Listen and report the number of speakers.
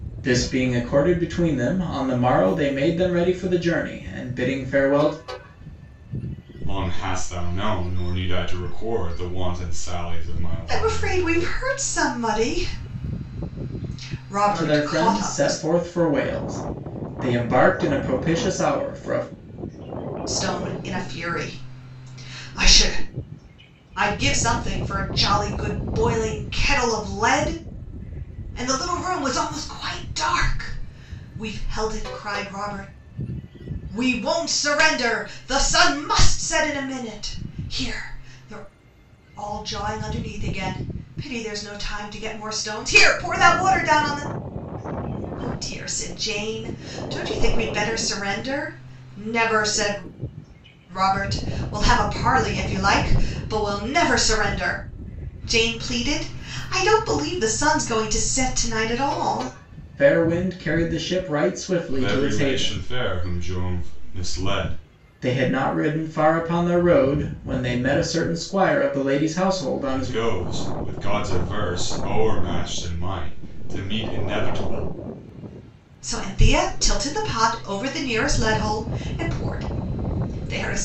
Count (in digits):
3